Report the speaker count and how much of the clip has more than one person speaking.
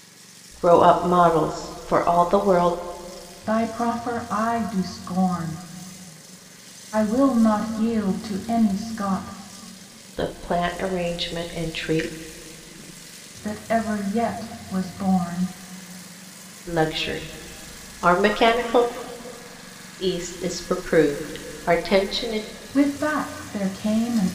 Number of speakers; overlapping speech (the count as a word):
two, no overlap